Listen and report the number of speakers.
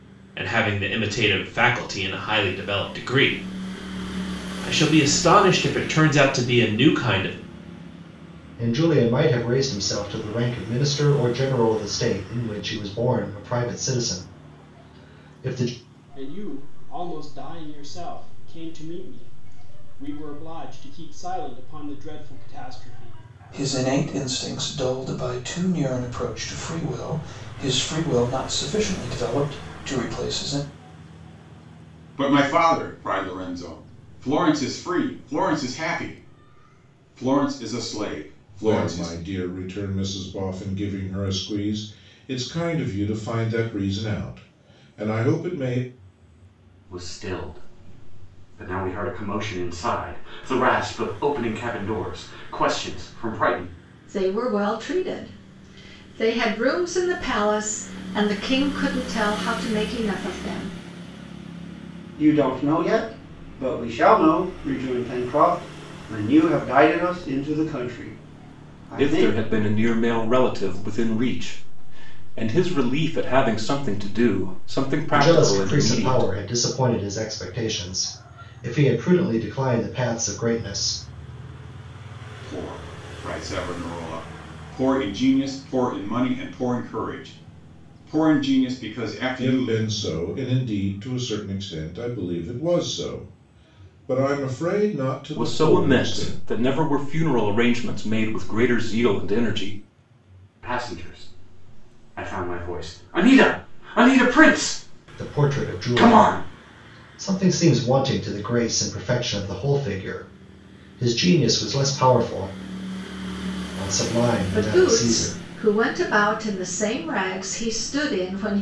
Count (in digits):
10